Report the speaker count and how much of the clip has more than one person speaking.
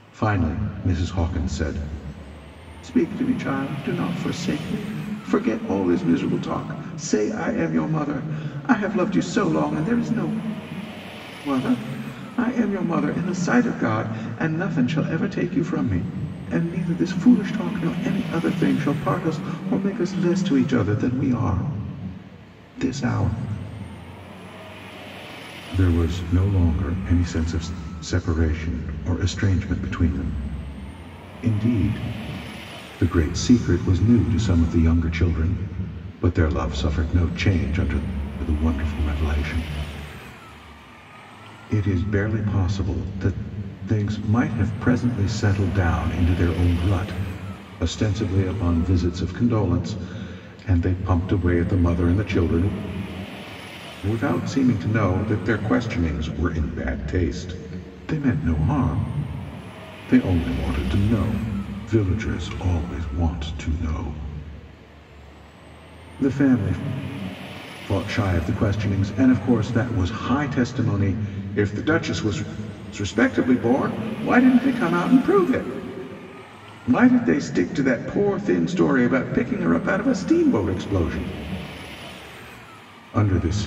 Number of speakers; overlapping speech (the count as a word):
one, no overlap